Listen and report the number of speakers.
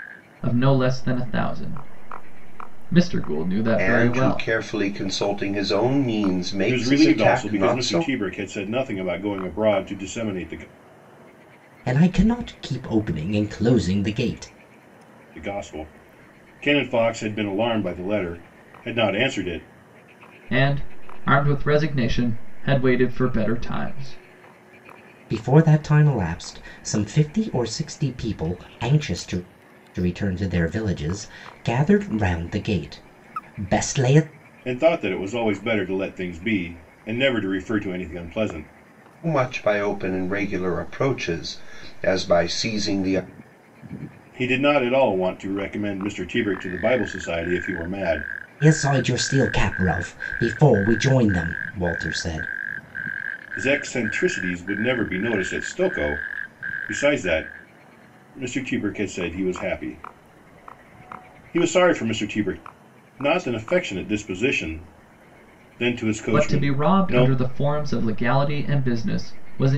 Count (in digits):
4